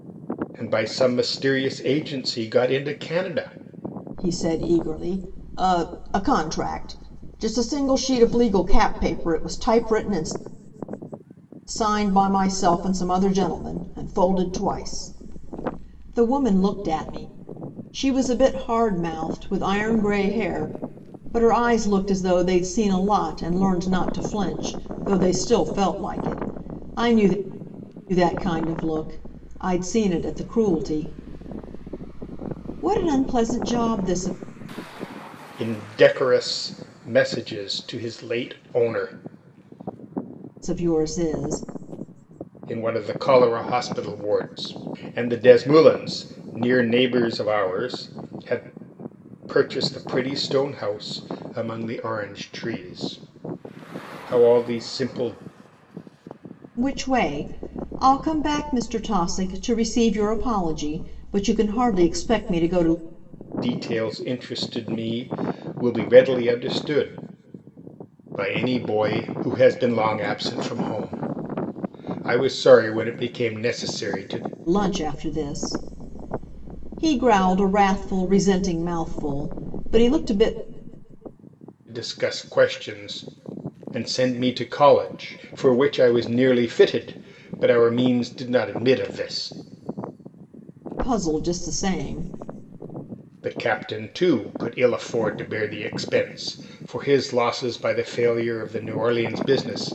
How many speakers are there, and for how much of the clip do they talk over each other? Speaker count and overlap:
2, no overlap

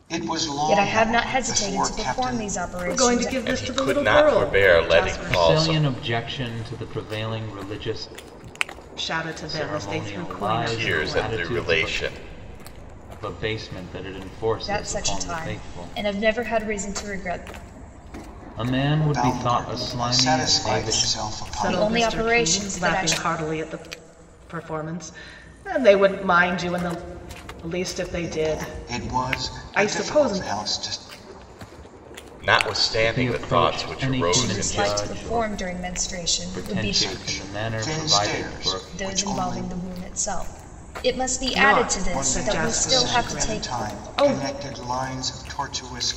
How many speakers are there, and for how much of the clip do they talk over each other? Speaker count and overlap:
5, about 51%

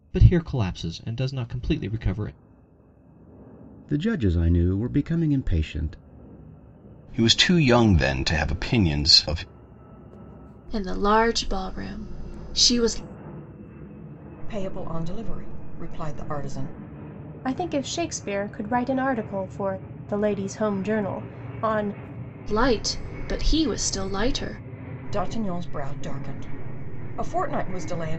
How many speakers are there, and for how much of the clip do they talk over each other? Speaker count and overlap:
6, no overlap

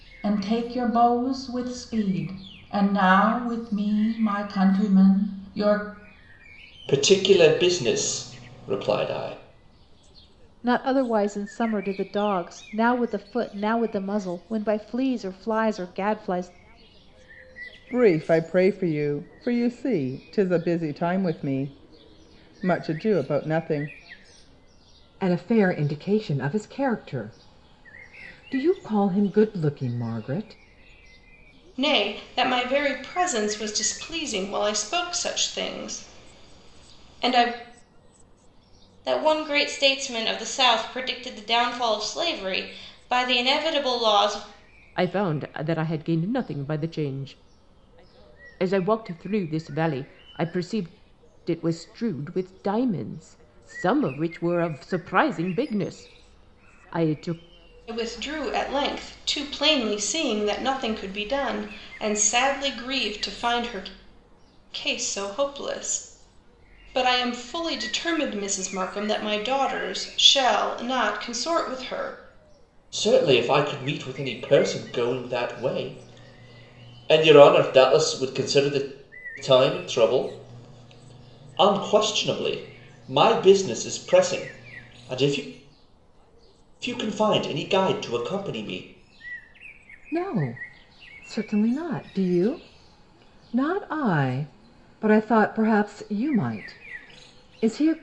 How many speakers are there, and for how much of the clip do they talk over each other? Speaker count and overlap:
8, no overlap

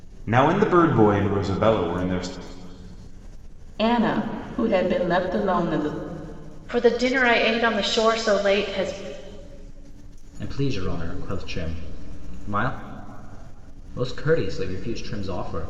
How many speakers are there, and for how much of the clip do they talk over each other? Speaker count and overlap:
4, no overlap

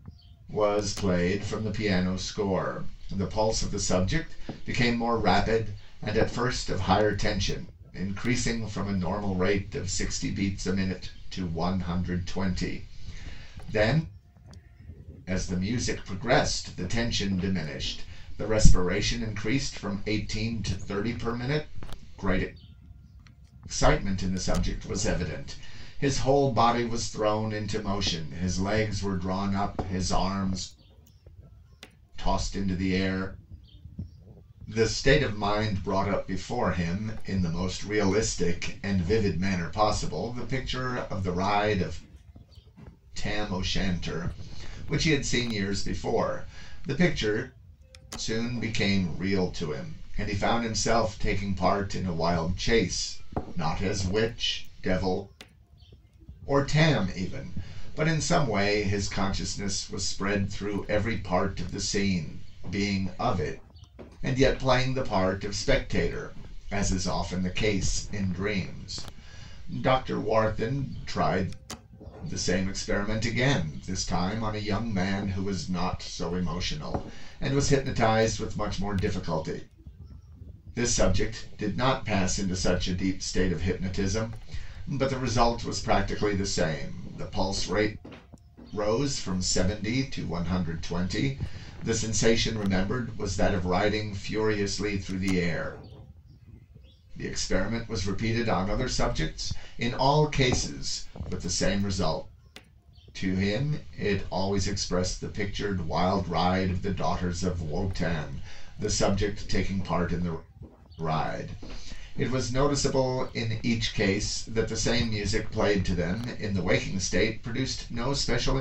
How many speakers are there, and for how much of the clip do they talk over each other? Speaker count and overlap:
1, no overlap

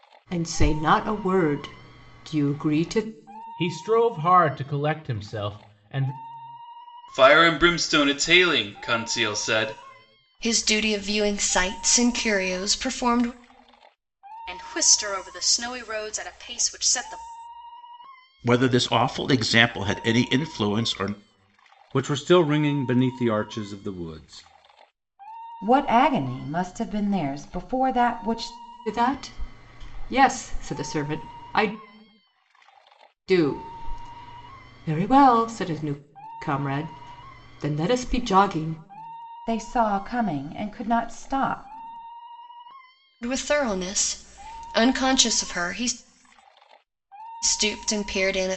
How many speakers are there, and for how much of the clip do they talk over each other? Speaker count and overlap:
8, no overlap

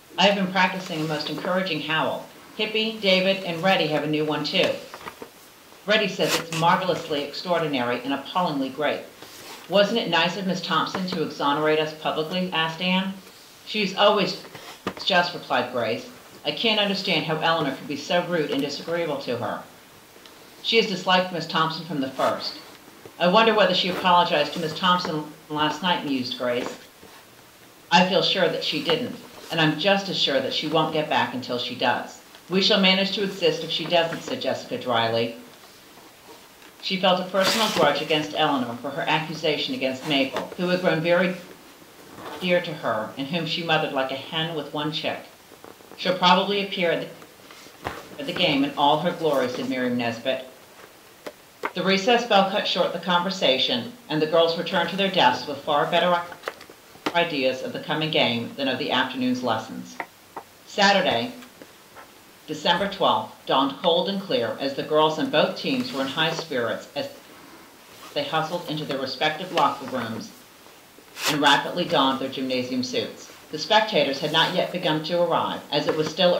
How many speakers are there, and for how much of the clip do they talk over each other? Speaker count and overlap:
1, no overlap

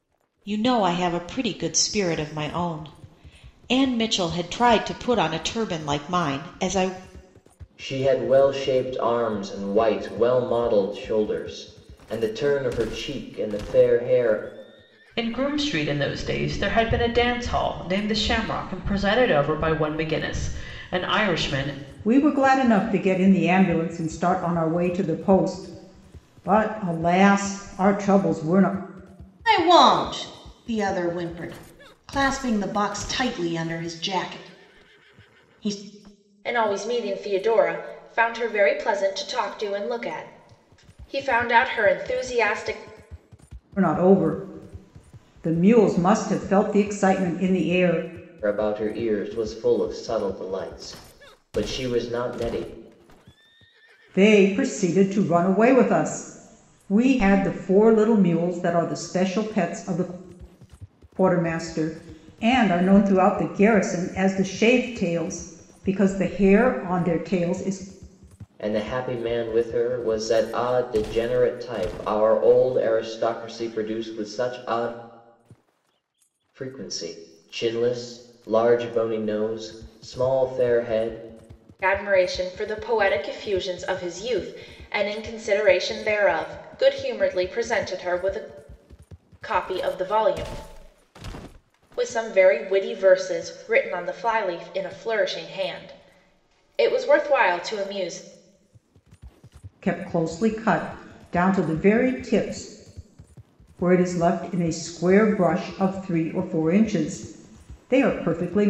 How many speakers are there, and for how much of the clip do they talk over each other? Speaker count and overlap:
6, no overlap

